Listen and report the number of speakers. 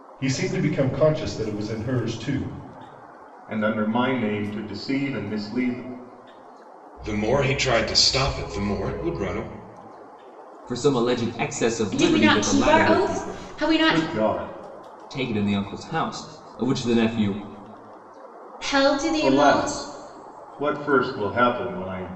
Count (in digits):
5